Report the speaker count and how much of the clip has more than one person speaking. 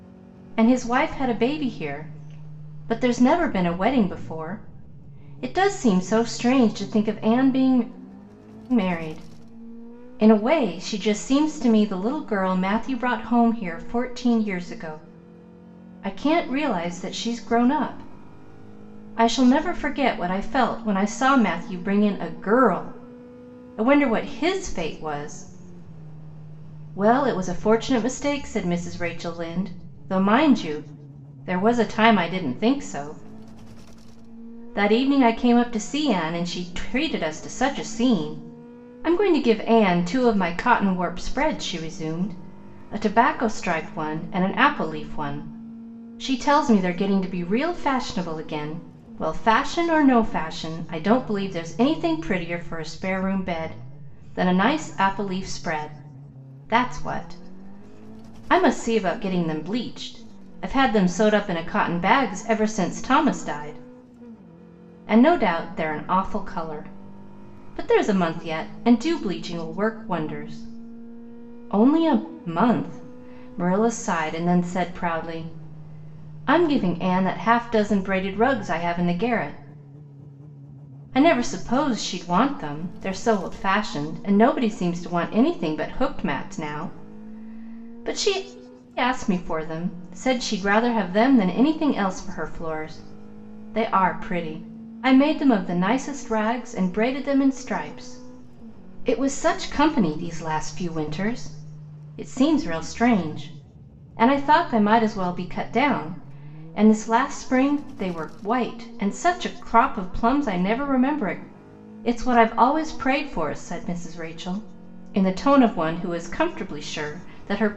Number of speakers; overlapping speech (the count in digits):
1, no overlap